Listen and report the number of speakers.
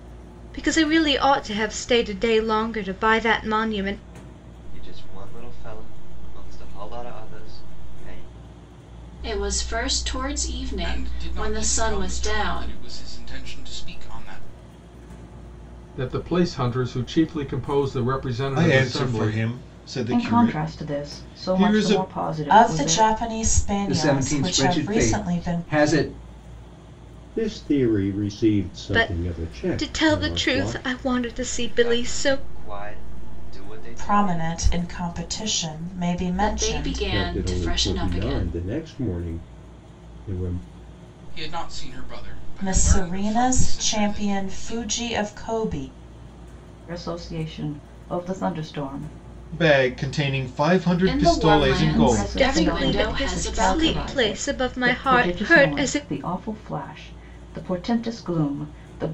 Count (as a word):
ten